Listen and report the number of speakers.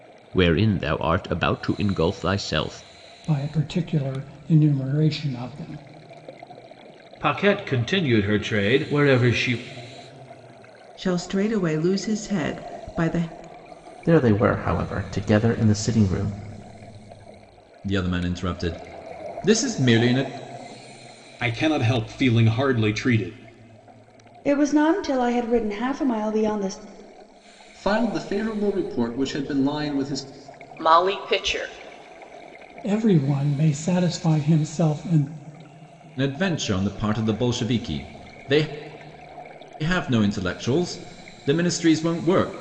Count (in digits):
10